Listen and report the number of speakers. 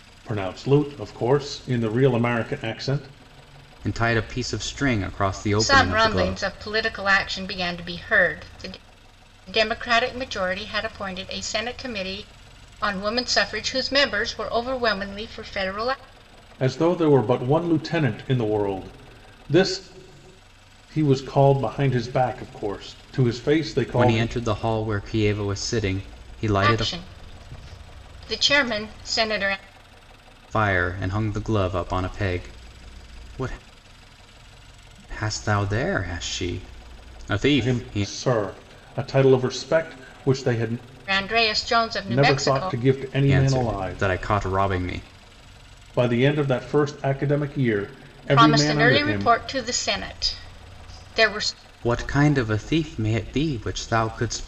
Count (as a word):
three